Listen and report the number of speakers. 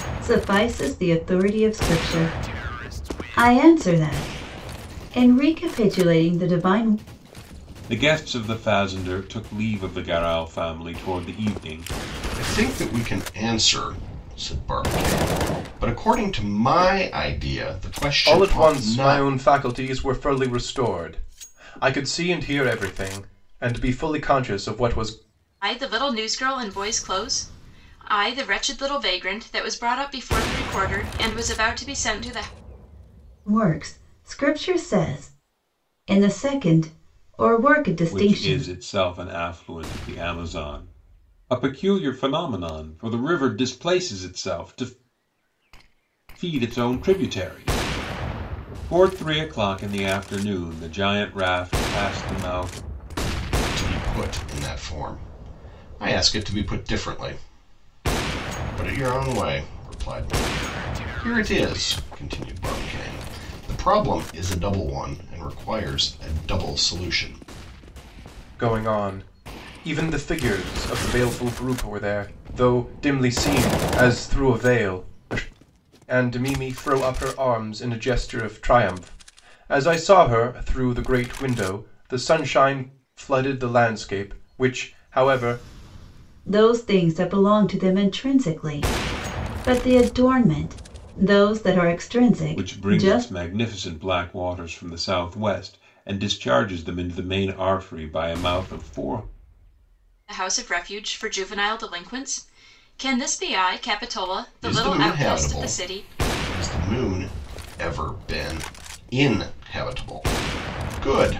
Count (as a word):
five